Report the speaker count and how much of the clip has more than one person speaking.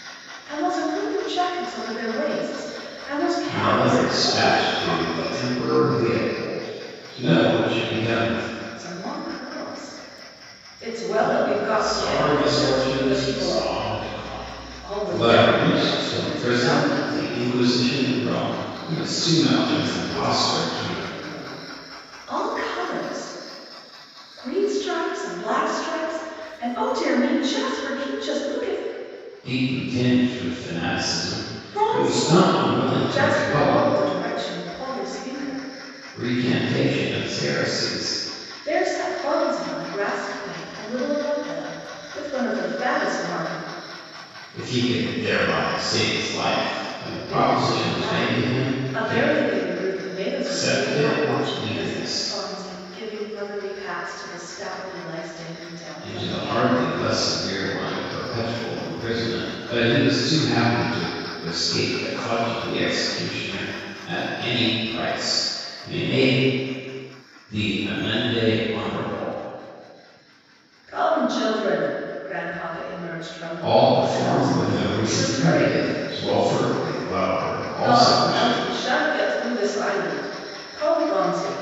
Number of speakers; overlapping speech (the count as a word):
two, about 23%